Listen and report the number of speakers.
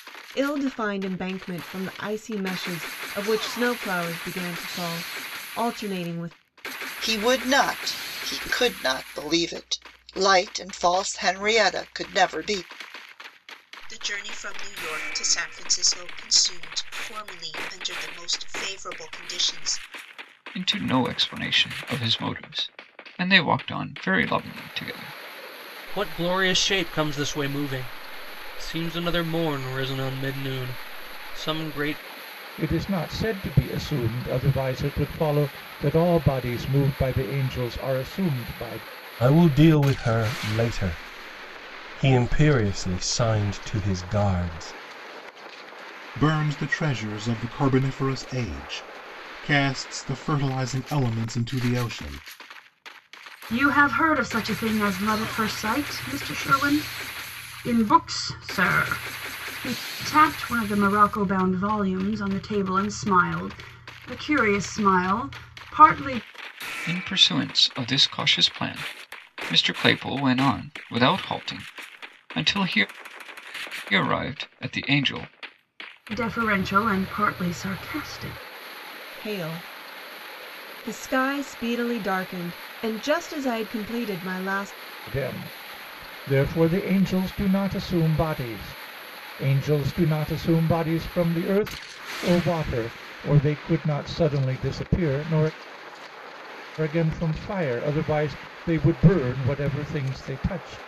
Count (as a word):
nine